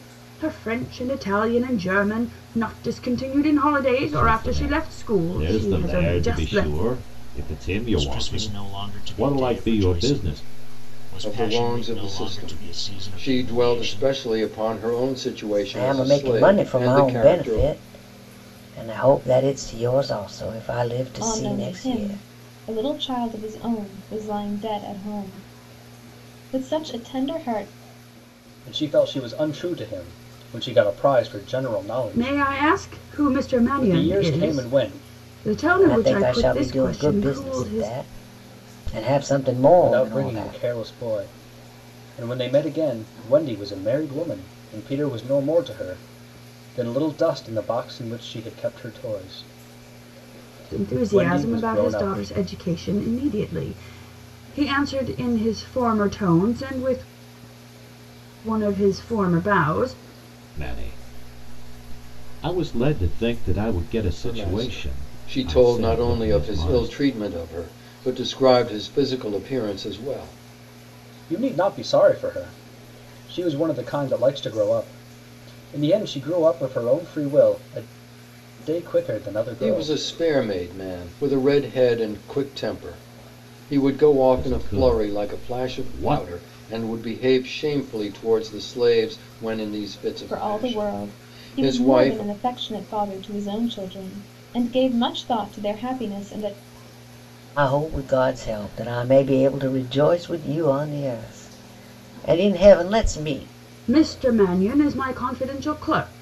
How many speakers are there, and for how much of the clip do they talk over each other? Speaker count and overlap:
7, about 25%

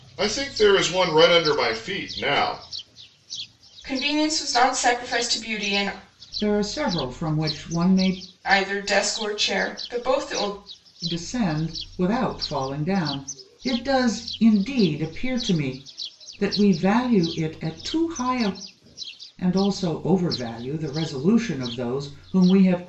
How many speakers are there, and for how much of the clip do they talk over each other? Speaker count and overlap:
3, no overlap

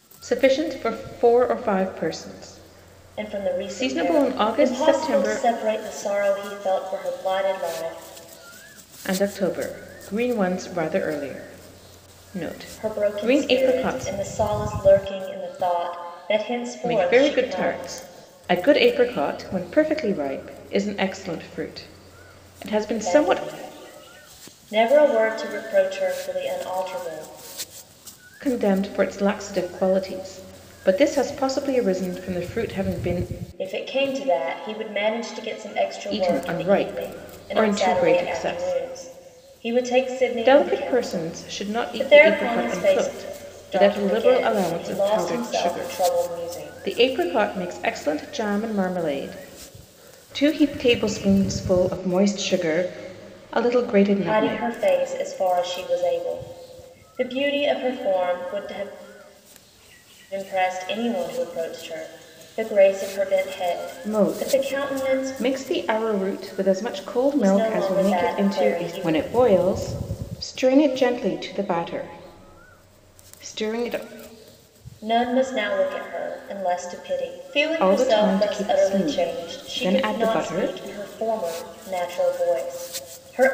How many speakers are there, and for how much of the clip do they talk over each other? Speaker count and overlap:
2, about 25%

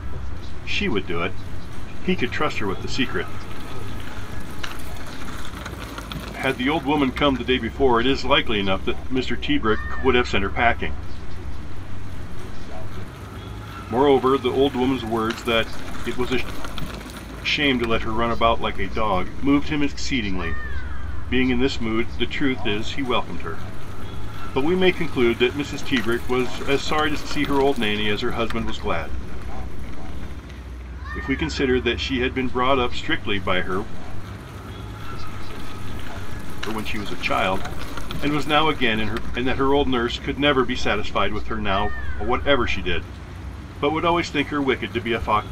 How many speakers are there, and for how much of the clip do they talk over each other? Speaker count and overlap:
2, about 53%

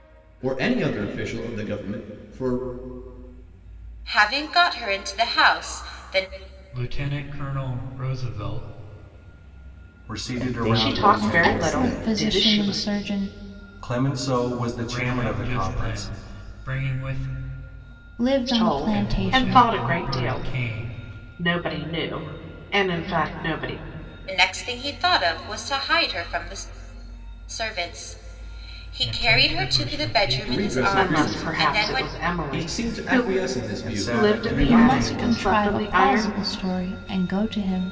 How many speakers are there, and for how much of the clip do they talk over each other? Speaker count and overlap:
7, about 33%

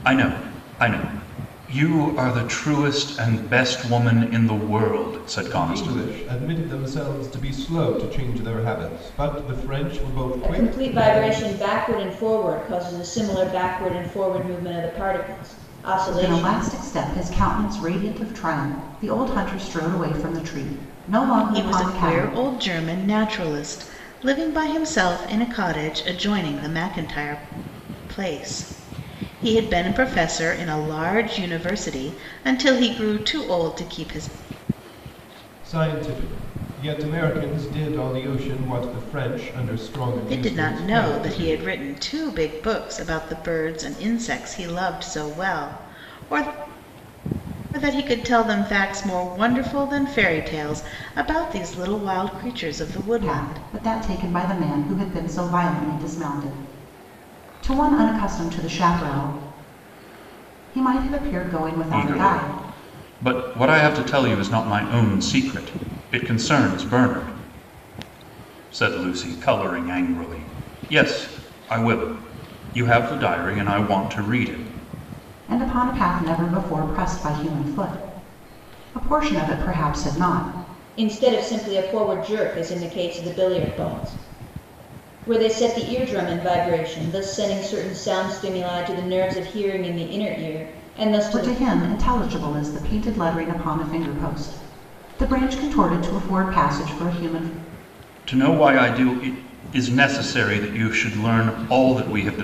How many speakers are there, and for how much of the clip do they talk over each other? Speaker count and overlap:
5, about 6%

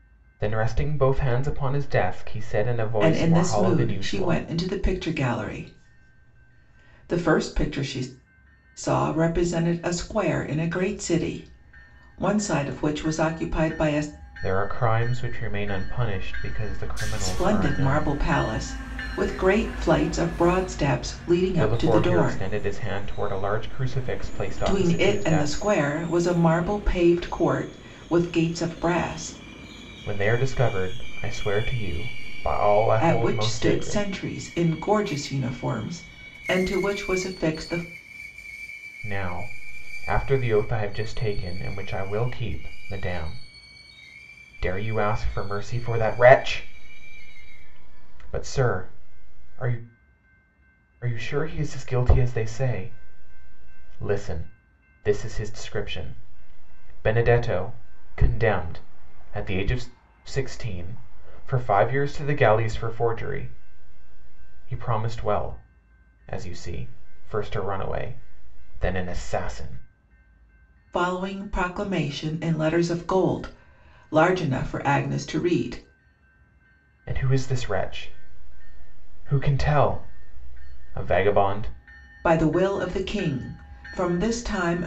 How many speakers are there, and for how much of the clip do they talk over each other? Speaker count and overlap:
2, about 7%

